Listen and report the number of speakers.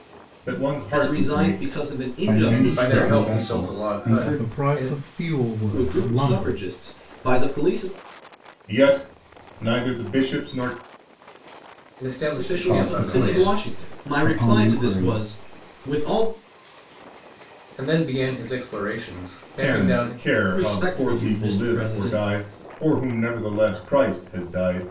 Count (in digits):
5